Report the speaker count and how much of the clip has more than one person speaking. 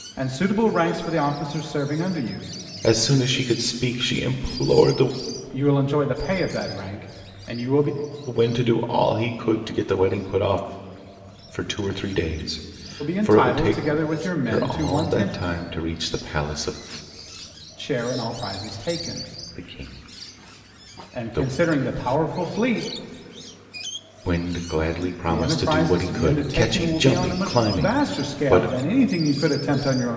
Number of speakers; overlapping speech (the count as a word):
two, about 19%